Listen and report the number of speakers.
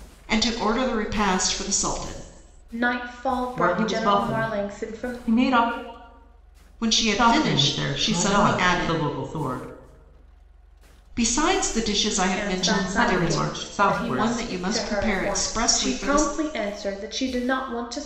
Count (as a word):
three